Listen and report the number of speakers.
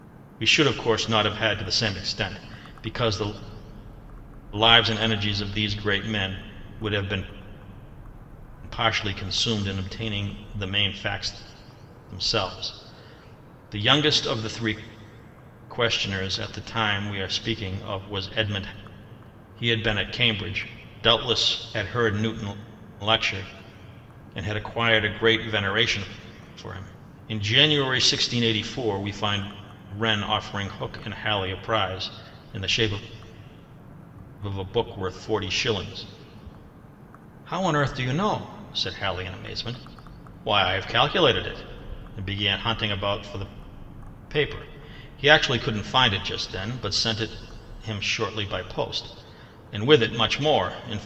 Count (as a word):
one